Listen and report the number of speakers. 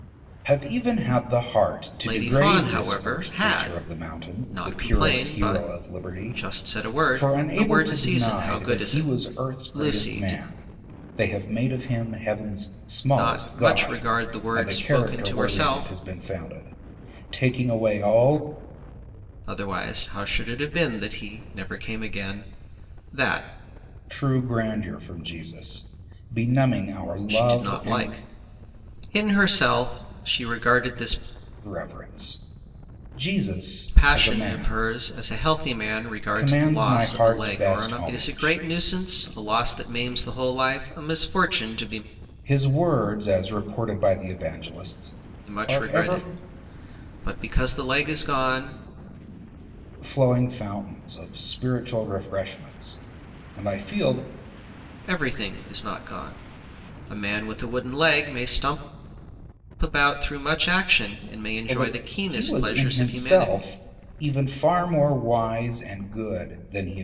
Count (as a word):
two